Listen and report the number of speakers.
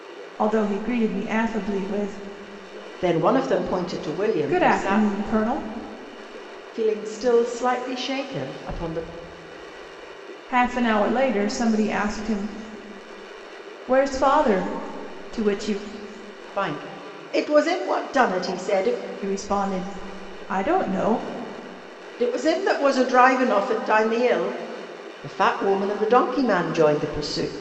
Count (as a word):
two